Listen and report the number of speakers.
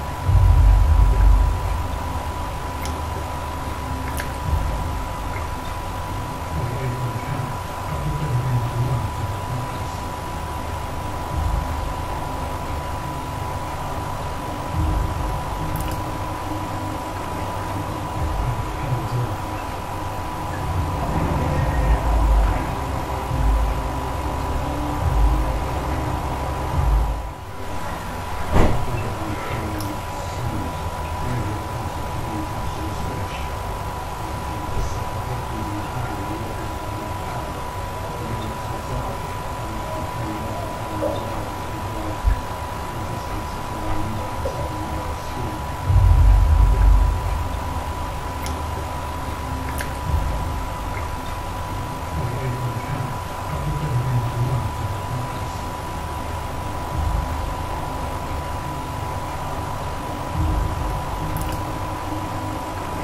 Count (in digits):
0